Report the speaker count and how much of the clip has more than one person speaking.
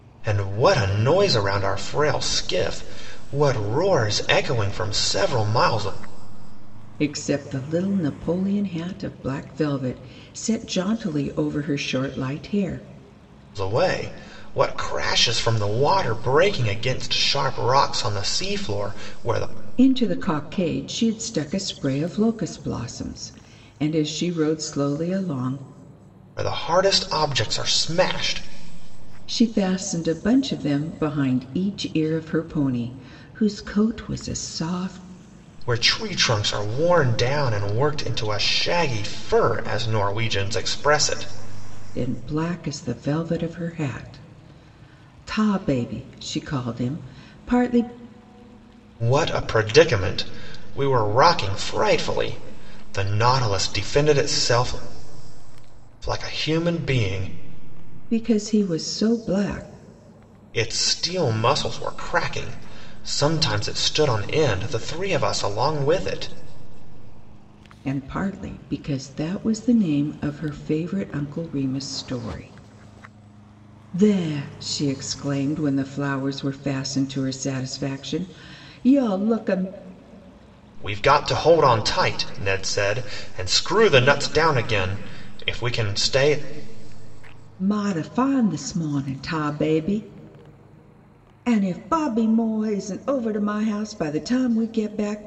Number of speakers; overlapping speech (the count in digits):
2, no overlap